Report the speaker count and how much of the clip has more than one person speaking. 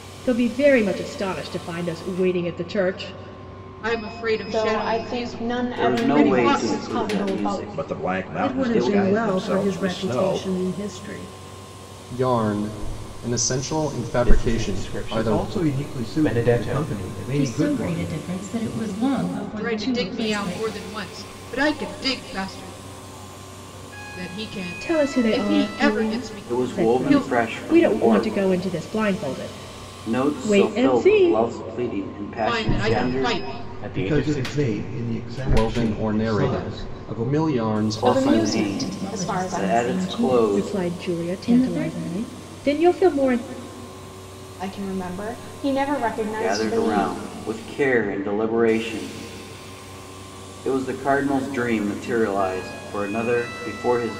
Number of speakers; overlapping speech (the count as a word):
ten, about 48%